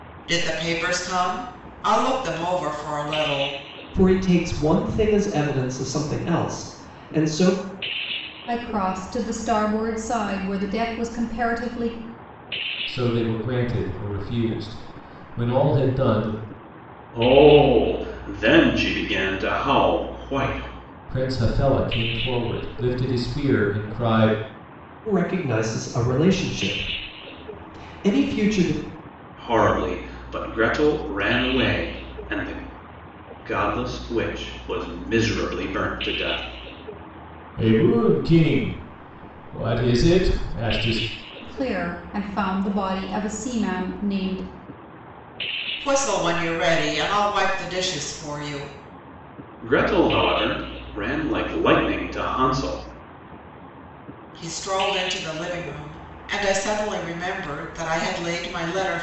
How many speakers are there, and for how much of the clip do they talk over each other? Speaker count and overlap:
5, no overlap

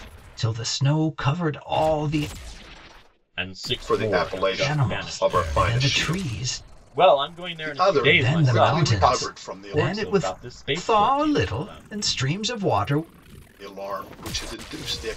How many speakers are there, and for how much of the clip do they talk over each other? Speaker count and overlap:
3, about 42%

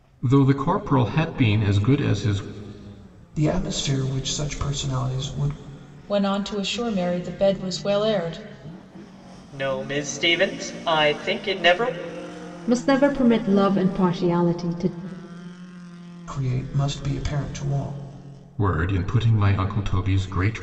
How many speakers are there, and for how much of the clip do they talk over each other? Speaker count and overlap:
5, no overlap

